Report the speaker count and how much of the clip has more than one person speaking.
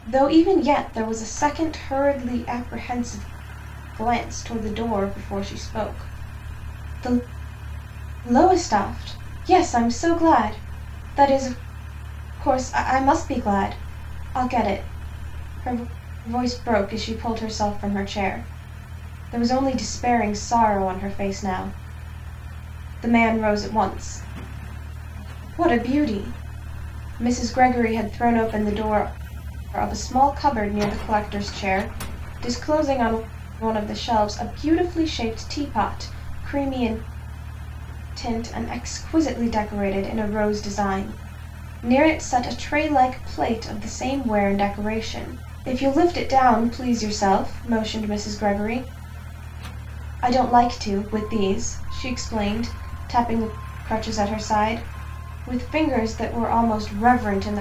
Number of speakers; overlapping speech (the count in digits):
1, no overlap